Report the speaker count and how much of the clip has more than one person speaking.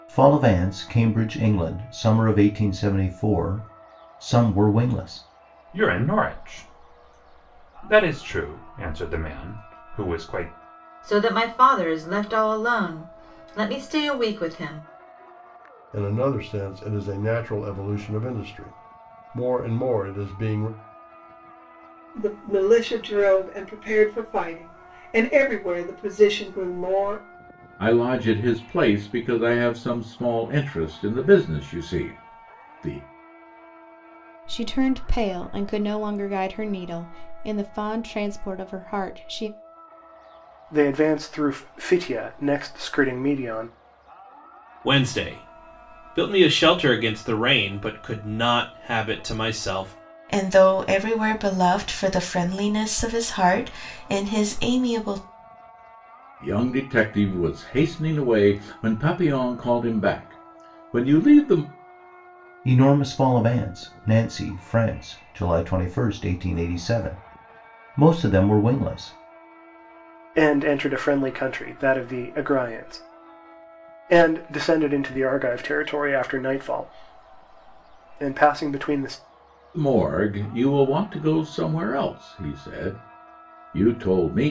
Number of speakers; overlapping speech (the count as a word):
ten, no overlap